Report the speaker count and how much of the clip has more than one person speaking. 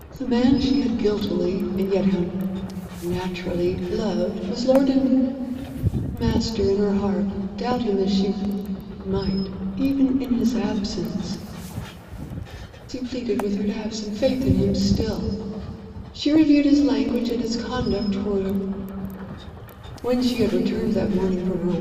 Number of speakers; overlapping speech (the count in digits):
1, no overlap